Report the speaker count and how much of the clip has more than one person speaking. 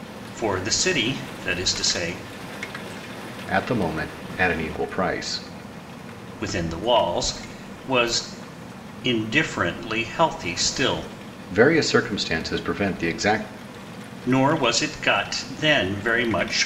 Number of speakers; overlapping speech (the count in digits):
2, no overlap